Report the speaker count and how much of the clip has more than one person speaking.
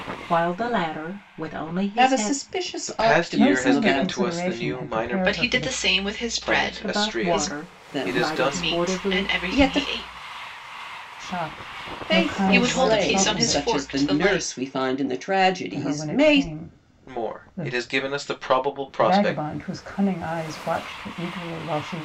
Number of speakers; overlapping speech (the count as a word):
five, about 53%